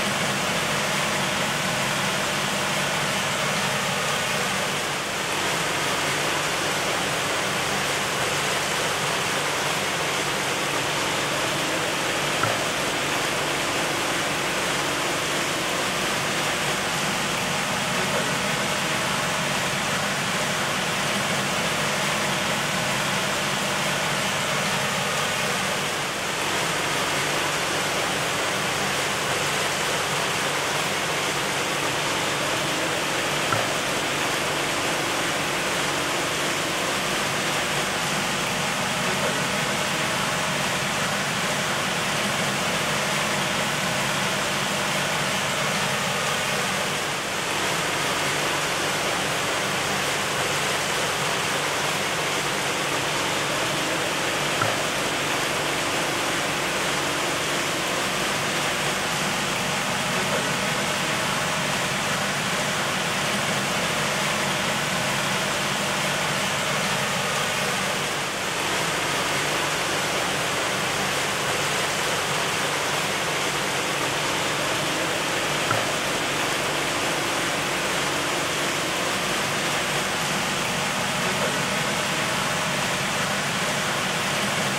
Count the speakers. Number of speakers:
zero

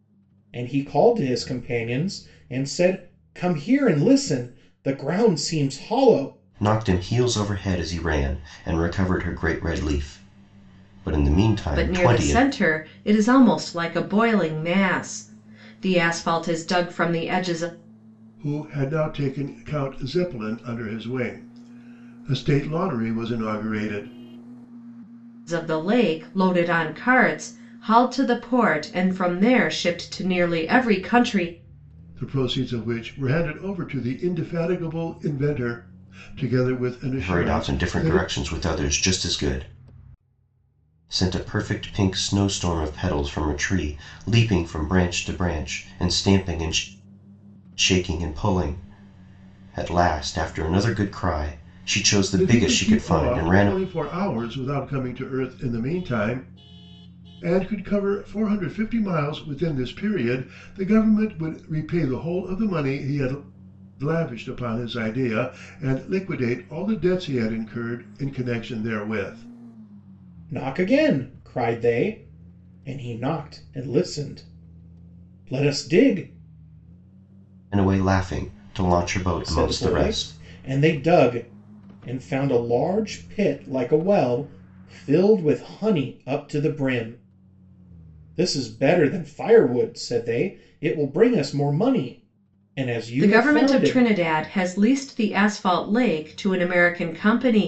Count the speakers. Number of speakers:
four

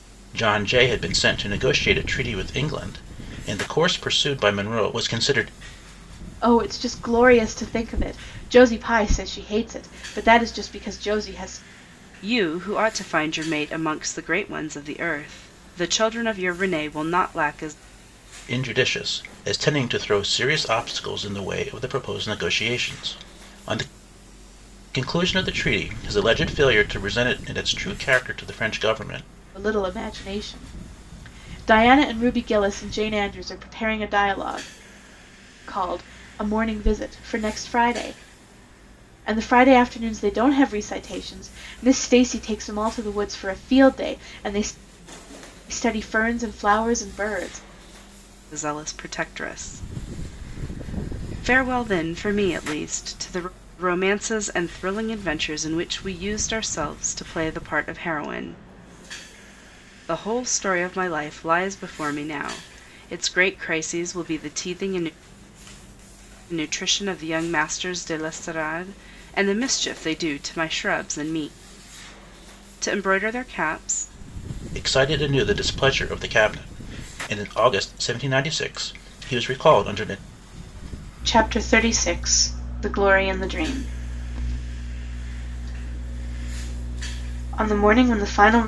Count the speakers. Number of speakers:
three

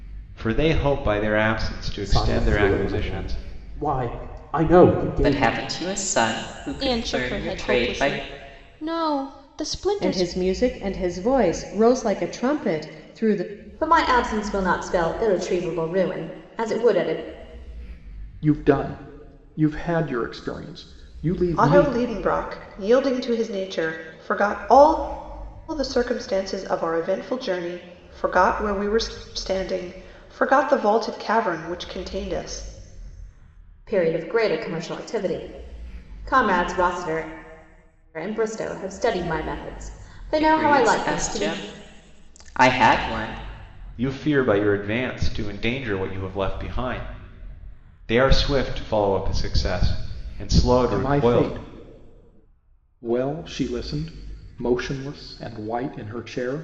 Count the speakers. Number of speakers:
eight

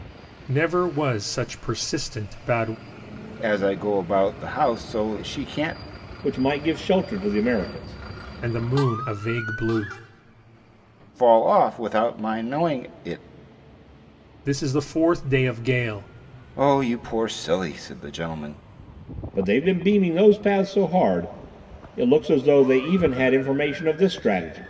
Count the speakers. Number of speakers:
three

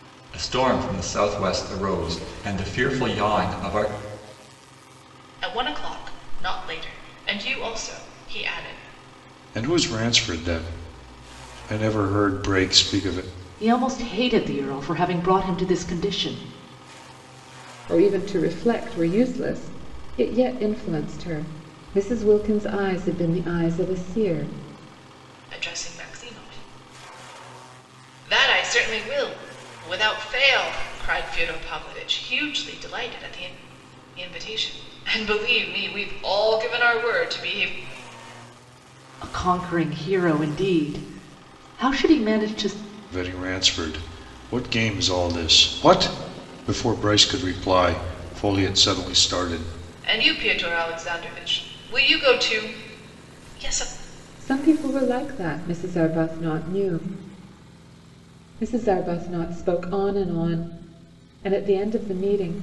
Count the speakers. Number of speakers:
five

